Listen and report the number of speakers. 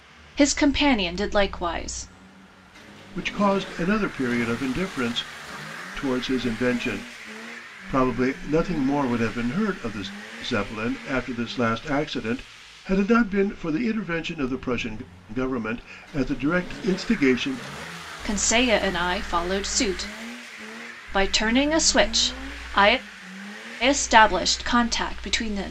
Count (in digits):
2